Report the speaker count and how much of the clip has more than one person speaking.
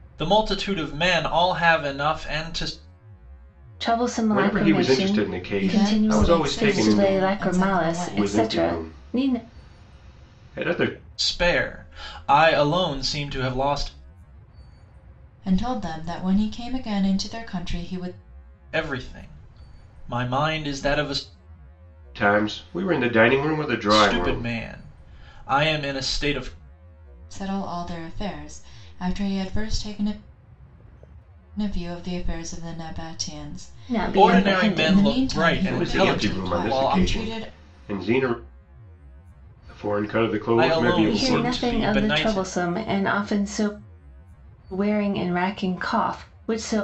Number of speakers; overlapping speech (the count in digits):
4, about 24%